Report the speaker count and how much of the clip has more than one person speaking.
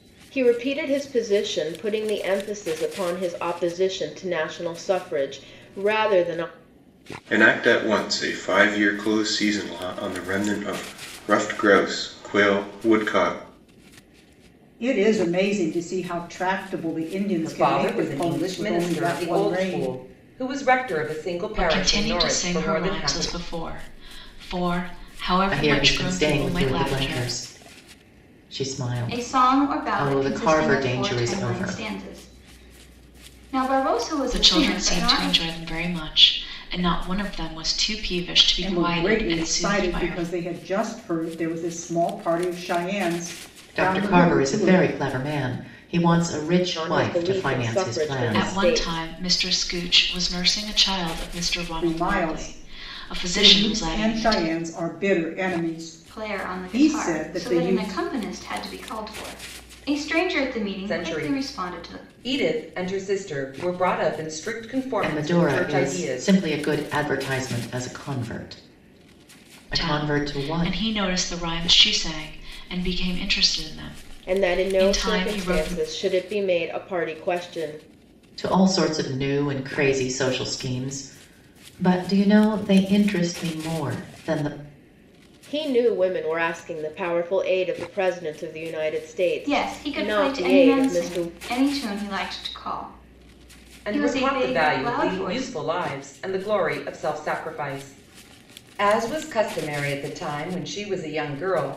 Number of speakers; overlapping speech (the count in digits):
7, about 29%